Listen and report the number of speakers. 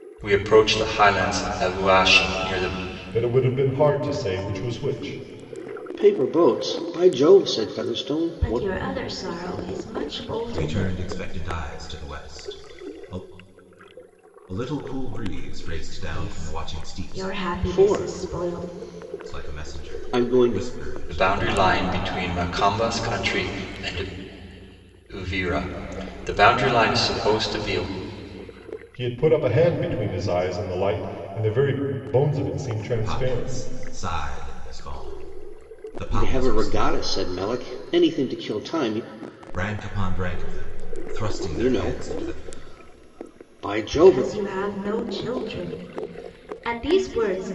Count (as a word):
five